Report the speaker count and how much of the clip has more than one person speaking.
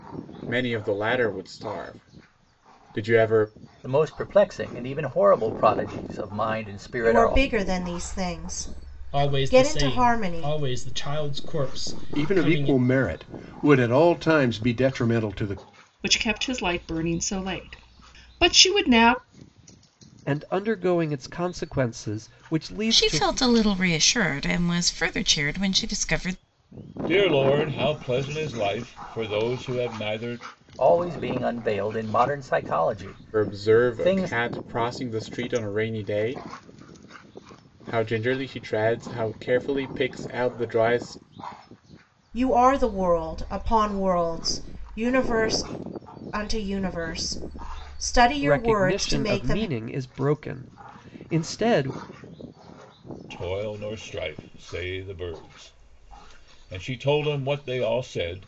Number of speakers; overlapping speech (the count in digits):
9, about 9%